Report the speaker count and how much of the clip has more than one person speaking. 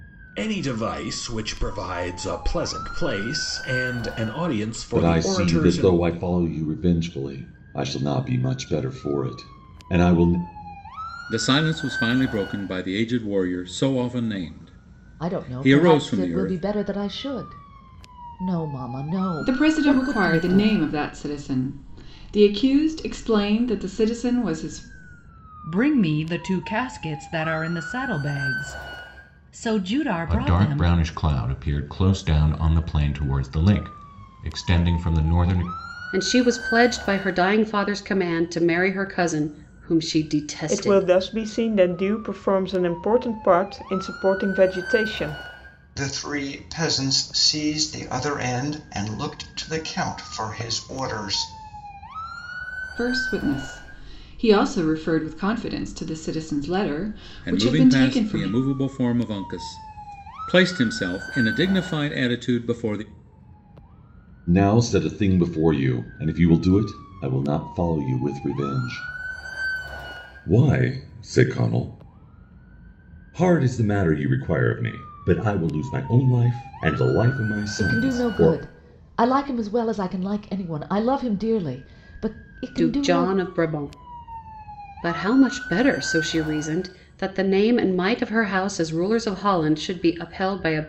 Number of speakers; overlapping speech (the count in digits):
10, about 8%